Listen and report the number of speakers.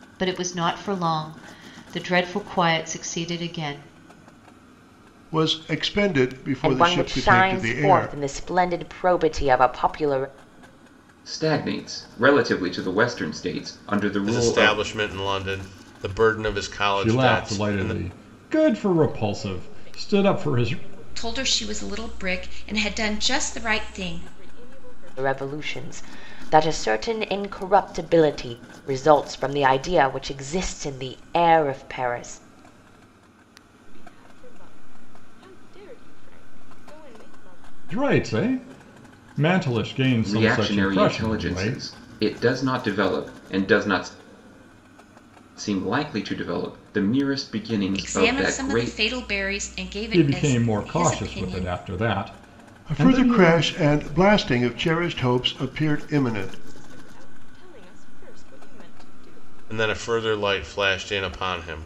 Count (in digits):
8